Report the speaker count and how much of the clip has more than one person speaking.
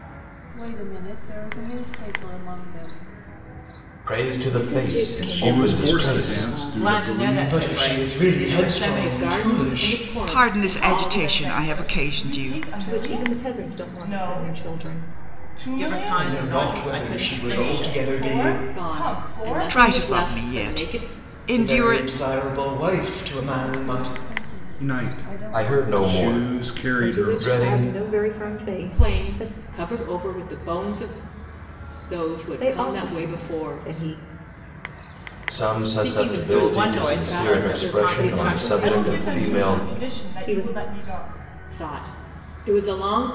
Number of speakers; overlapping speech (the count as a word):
ten, about 60%